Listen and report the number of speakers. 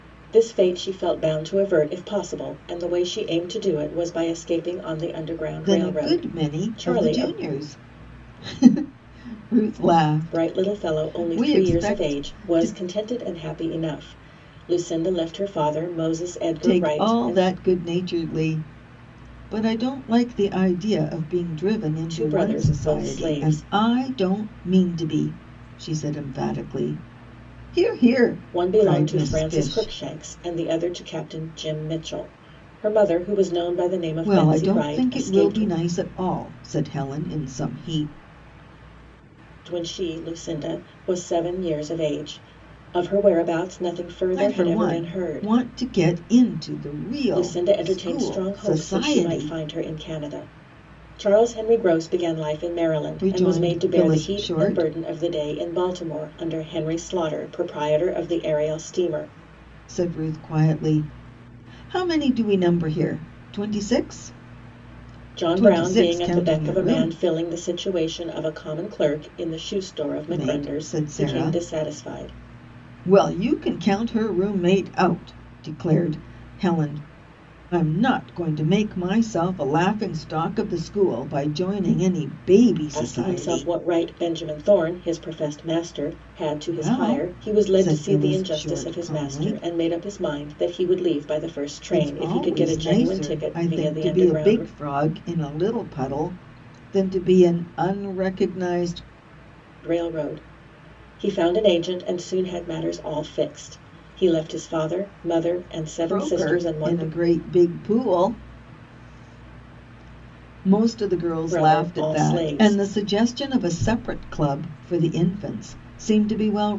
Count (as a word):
two